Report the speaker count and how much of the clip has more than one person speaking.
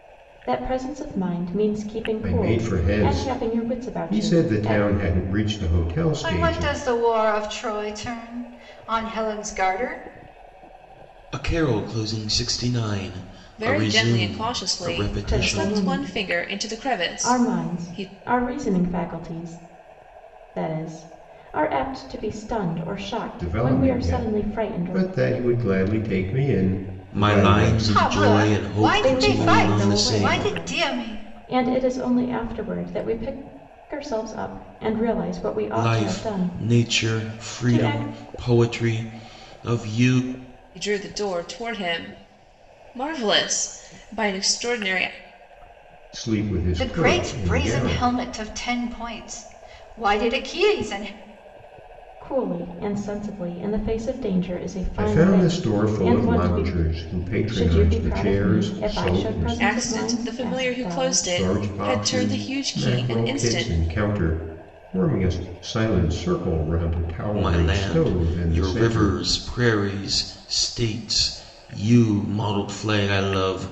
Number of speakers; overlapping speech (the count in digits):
5, about 37%